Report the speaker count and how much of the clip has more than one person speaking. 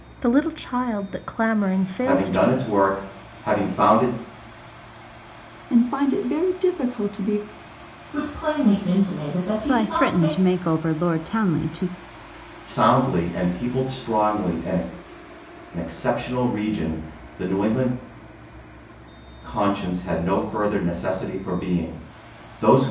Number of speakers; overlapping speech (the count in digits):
5, about 6%